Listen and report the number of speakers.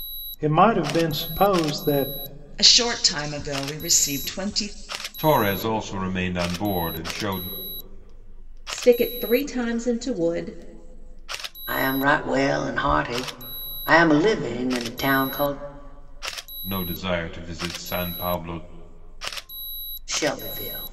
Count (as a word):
five